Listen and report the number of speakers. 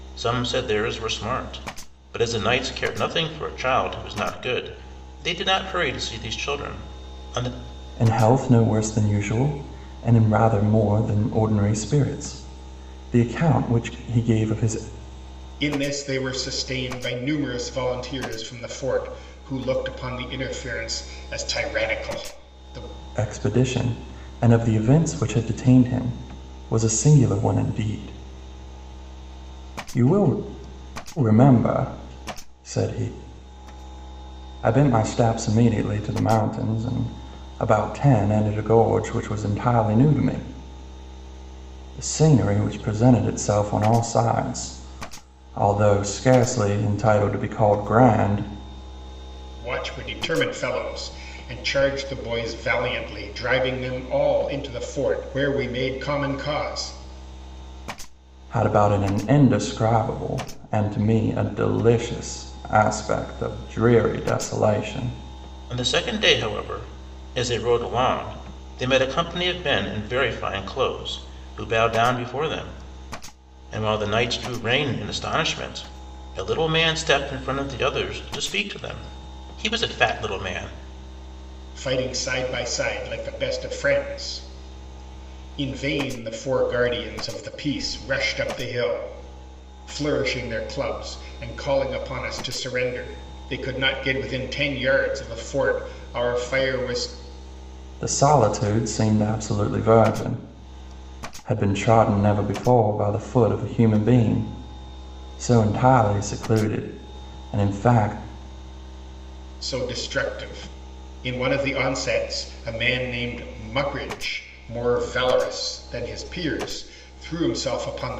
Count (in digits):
3